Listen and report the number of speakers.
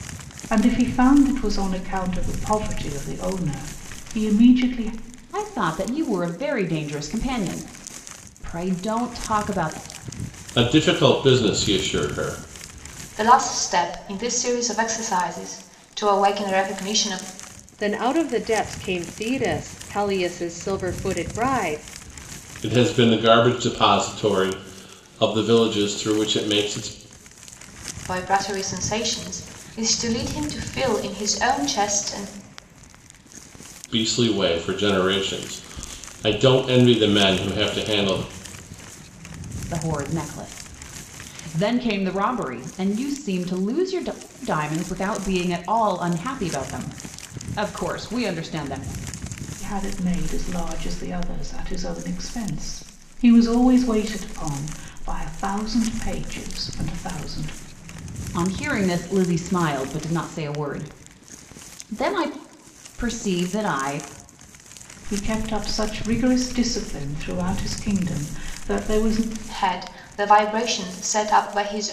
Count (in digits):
5